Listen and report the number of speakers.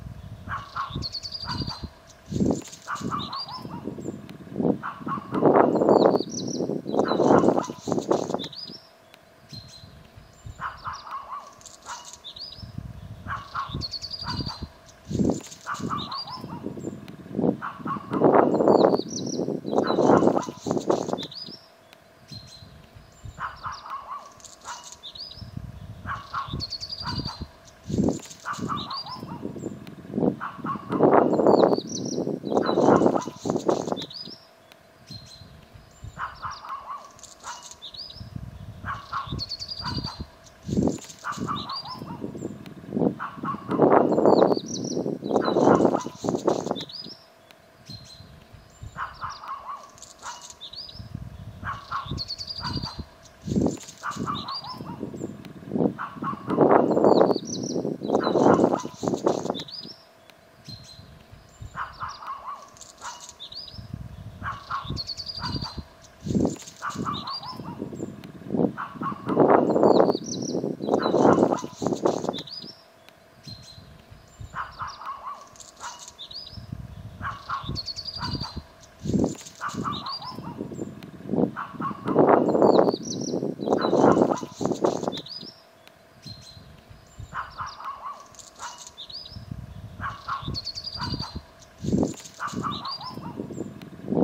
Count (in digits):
0